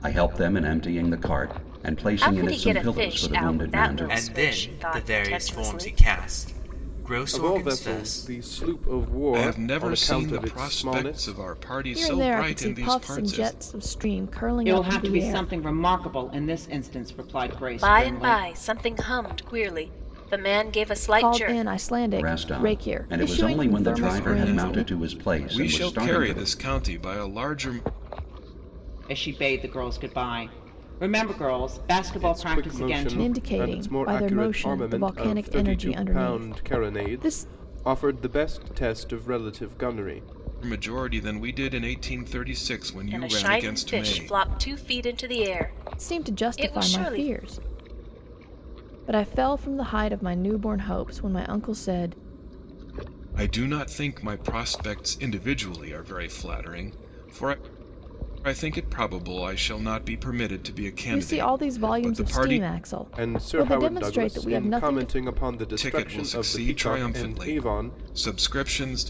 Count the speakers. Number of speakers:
seven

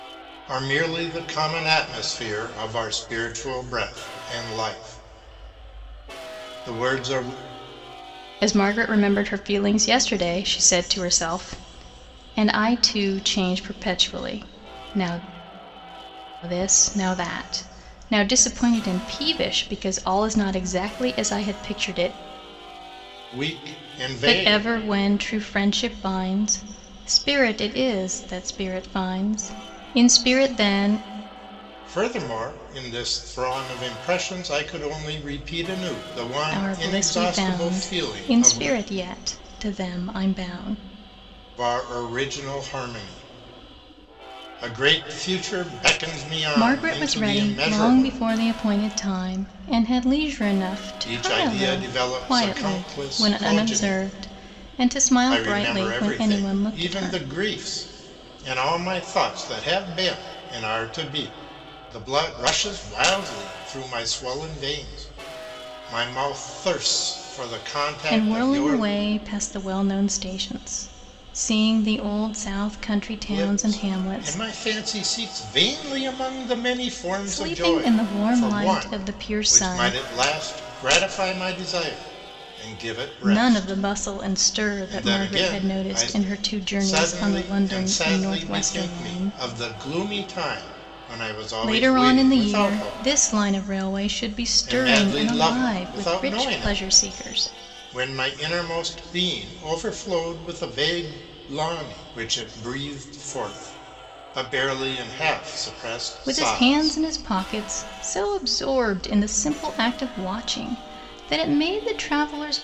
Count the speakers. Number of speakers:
two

